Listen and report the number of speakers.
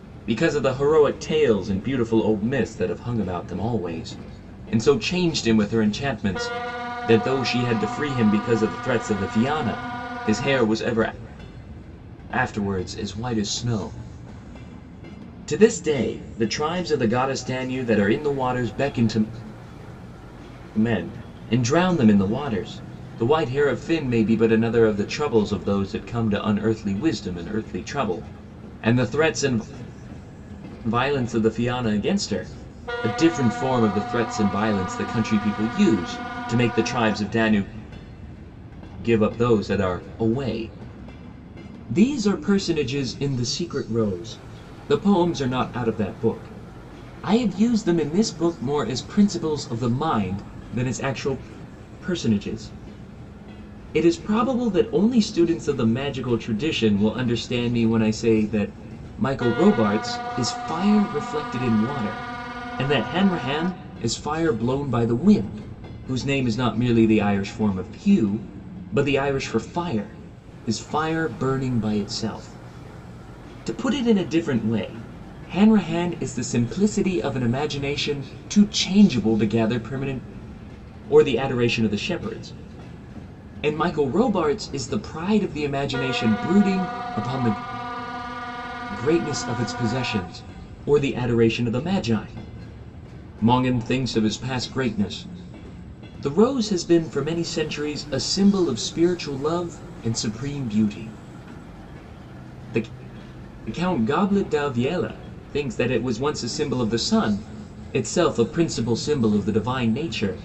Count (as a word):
one